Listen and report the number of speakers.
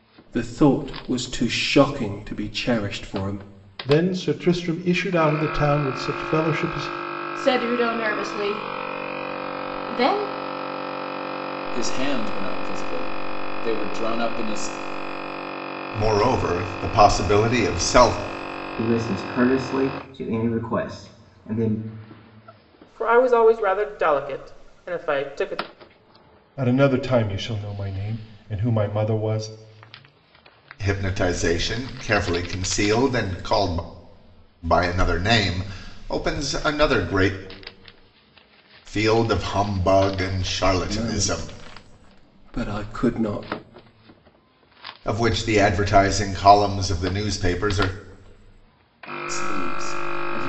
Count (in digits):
8